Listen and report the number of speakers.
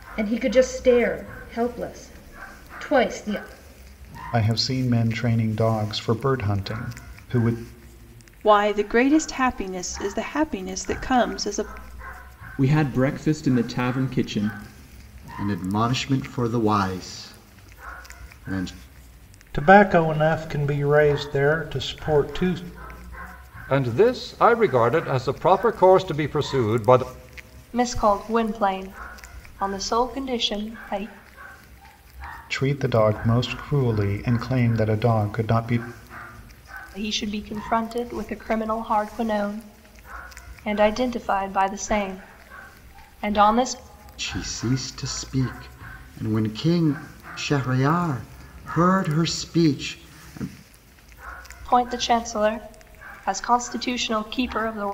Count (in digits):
8